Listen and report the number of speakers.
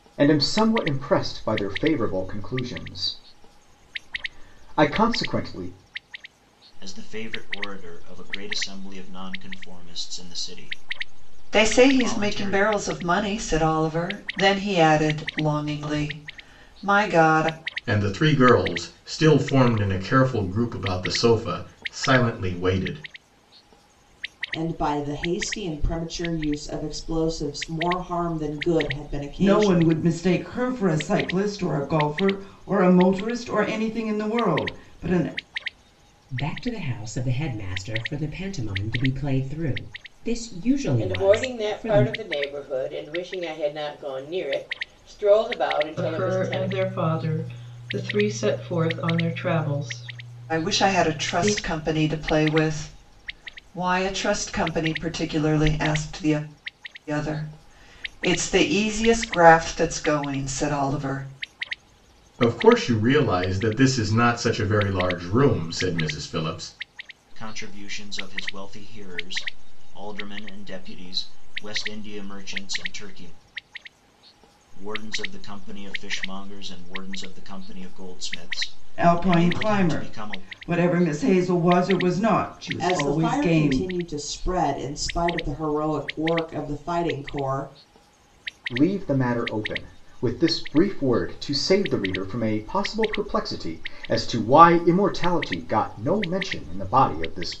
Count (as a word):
nine